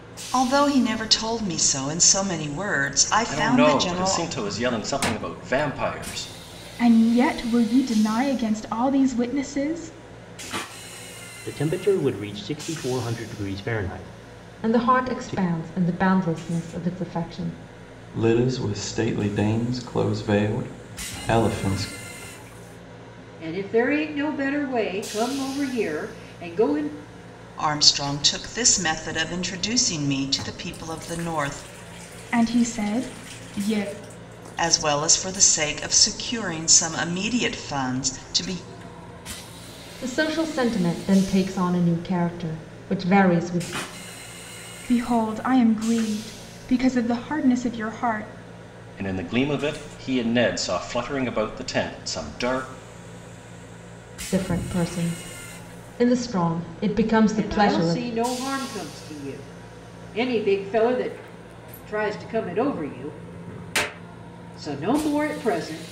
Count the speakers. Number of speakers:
seven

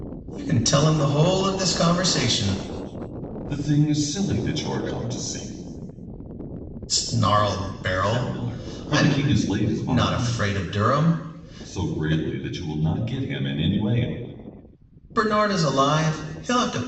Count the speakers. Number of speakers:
two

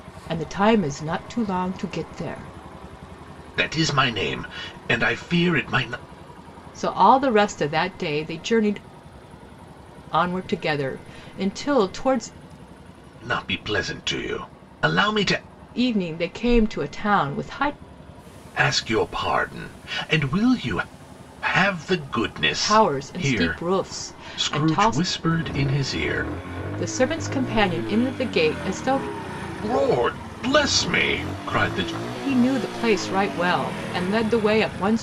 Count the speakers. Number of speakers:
two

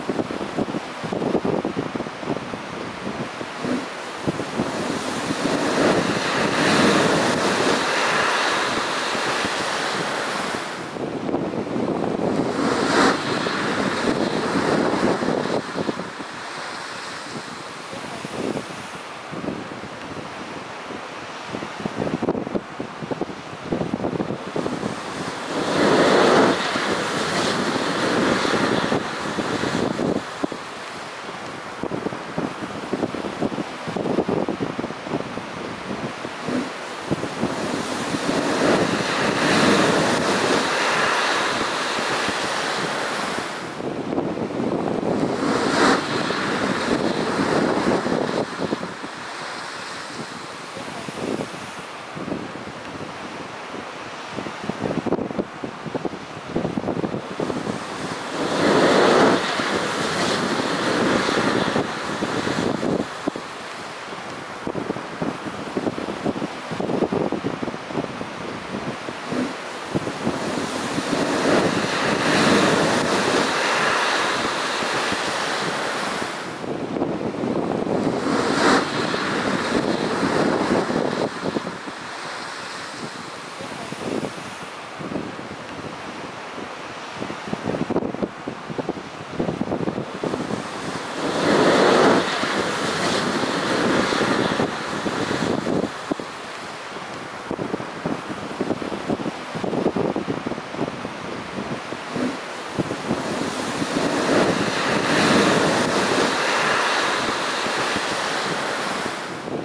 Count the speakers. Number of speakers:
zero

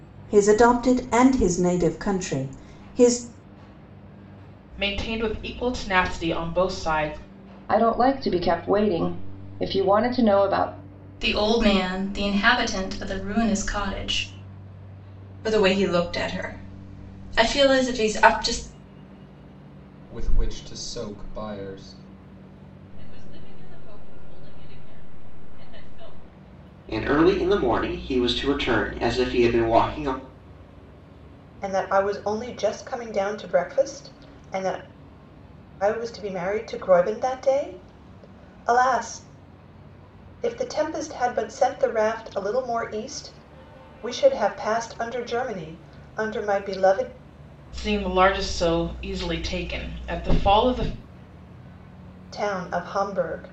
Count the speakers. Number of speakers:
nine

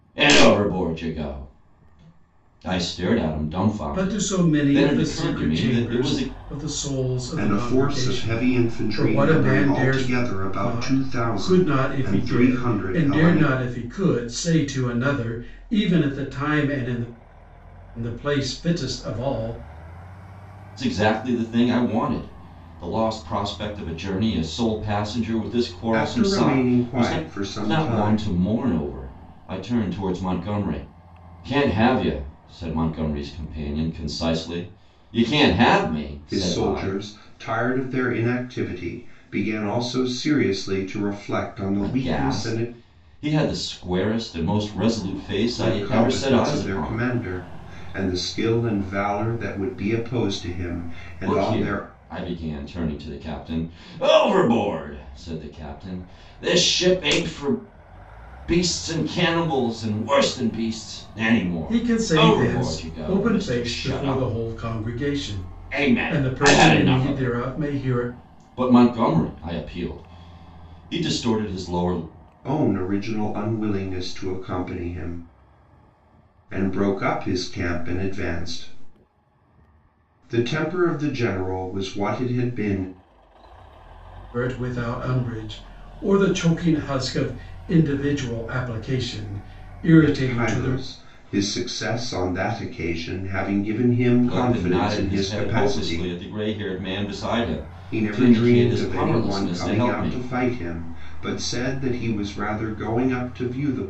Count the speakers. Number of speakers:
three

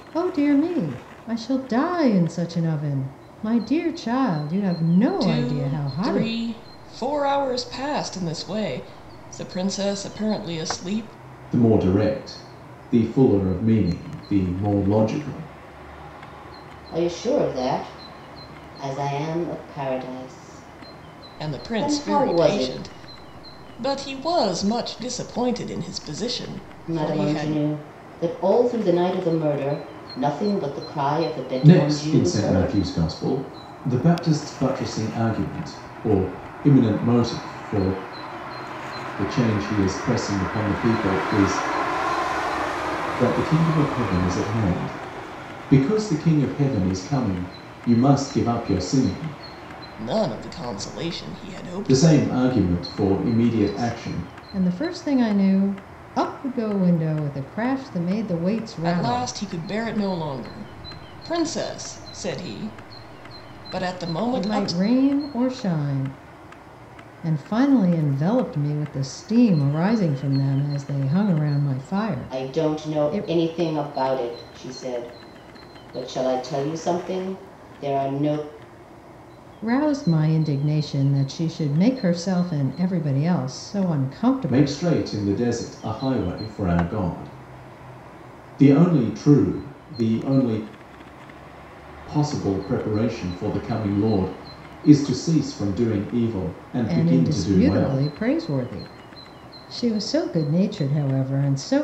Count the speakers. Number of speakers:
four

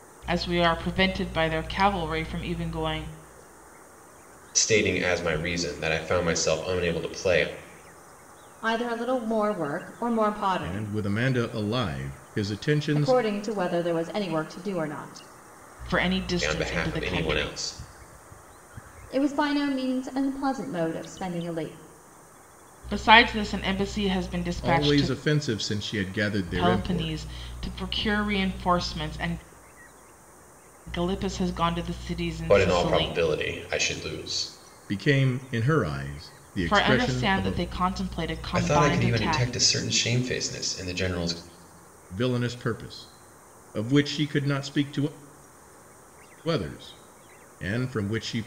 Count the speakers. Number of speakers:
four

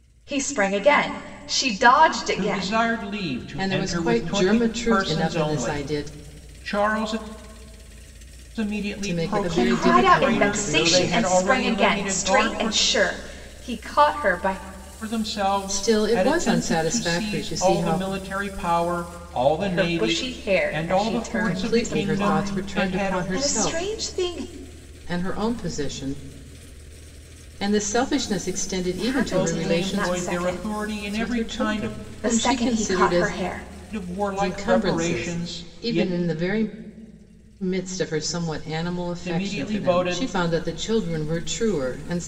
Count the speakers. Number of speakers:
three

